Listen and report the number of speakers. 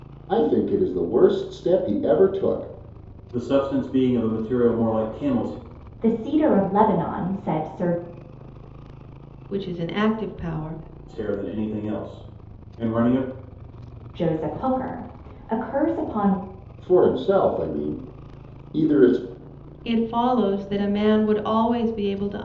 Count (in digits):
4